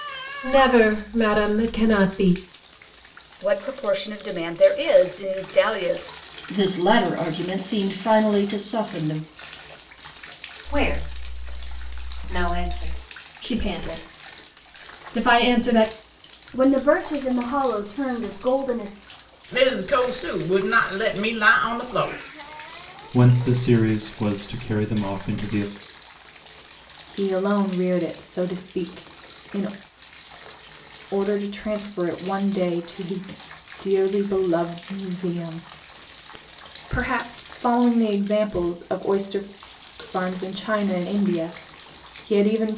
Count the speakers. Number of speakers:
9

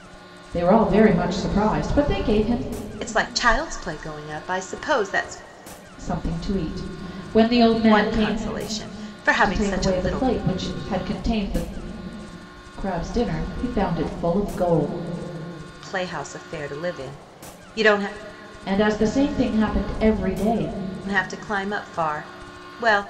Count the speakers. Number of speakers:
2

